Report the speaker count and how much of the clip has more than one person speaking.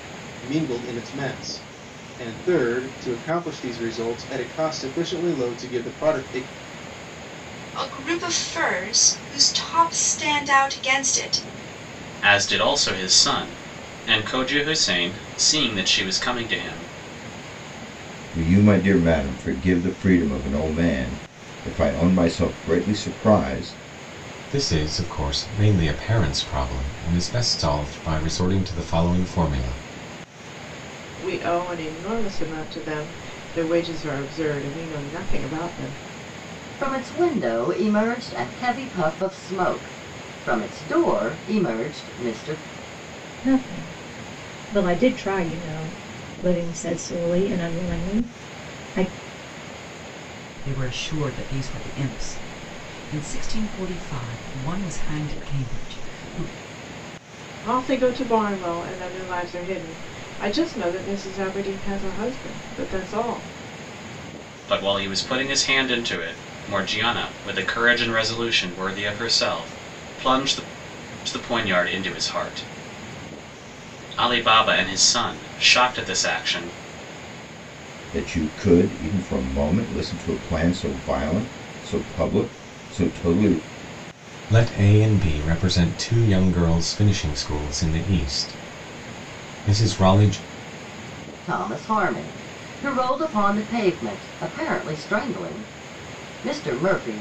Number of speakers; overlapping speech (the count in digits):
9, no overlap